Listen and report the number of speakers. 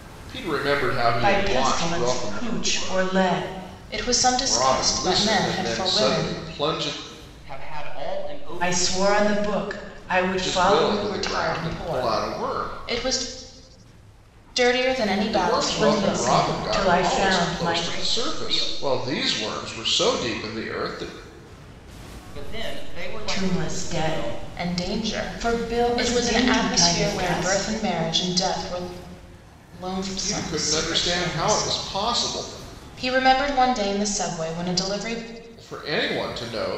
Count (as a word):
four